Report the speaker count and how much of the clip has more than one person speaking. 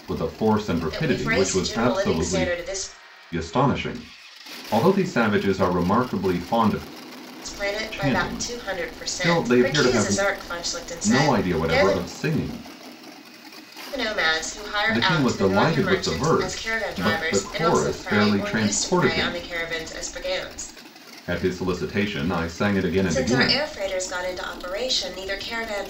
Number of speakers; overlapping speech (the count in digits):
2, about 39%